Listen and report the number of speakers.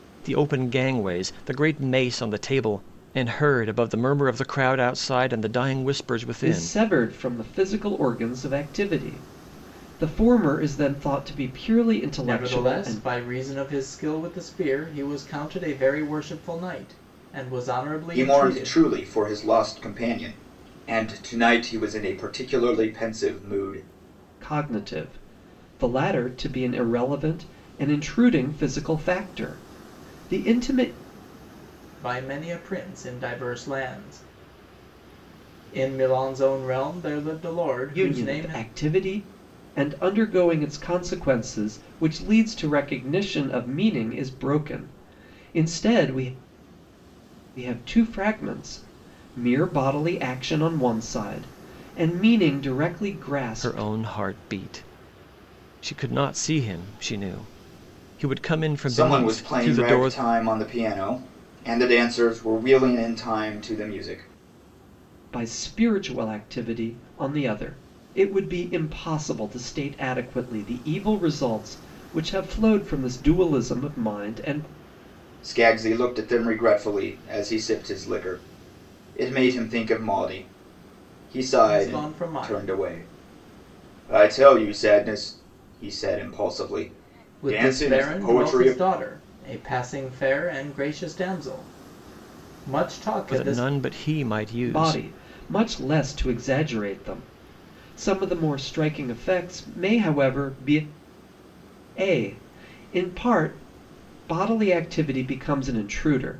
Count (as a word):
four